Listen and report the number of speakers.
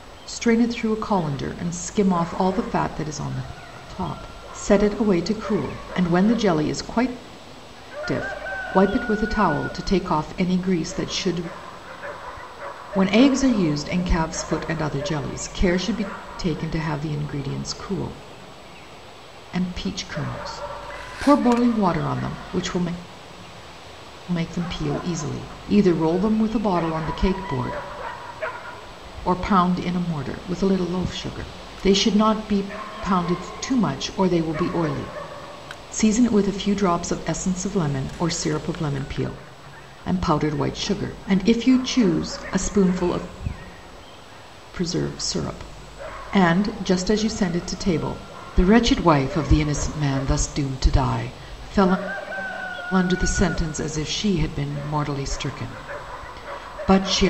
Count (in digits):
1